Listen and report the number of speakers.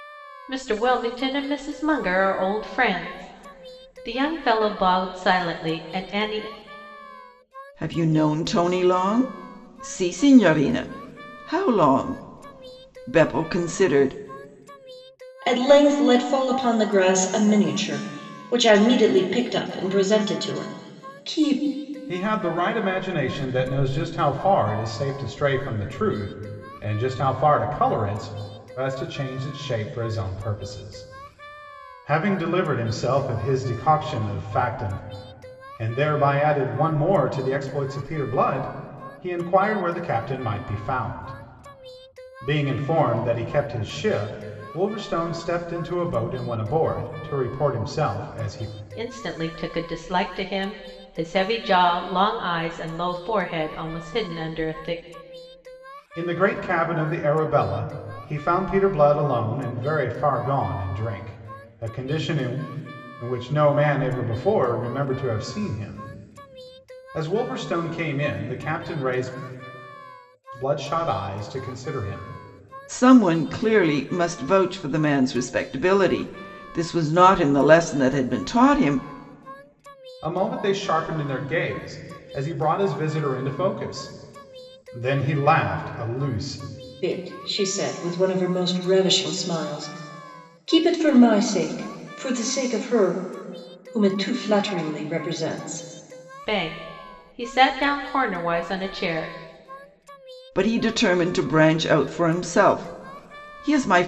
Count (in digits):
4